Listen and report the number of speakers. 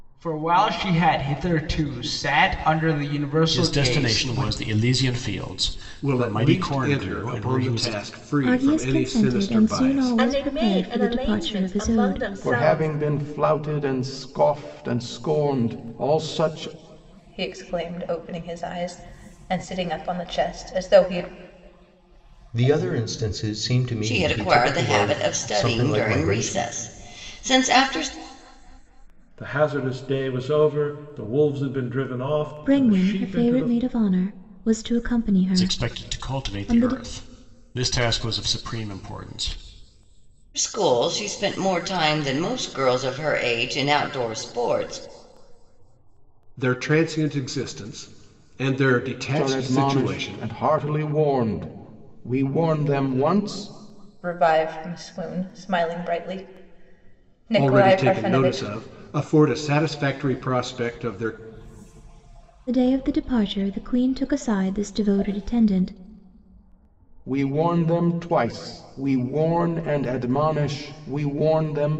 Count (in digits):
10